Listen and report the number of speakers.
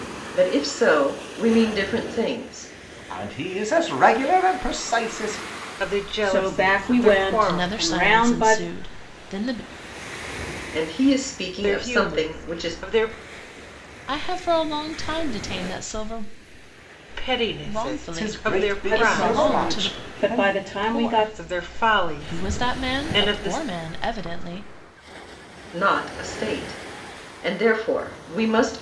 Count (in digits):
5